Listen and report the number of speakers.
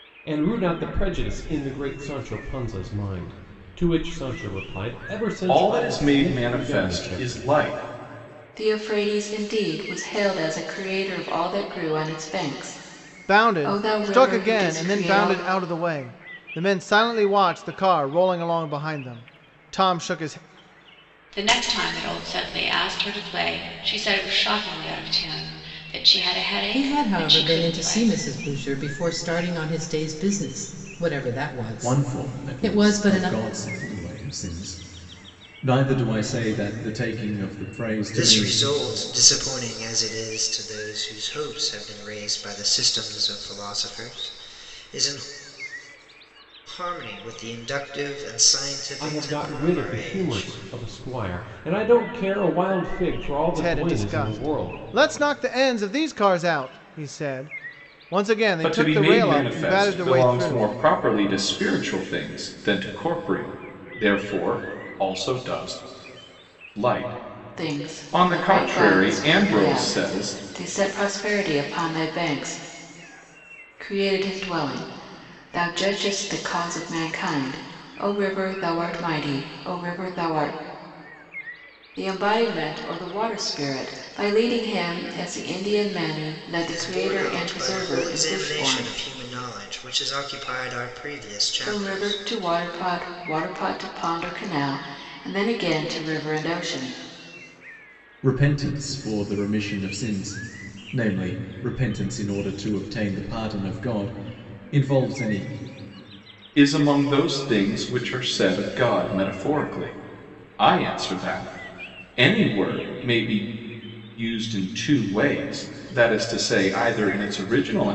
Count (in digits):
8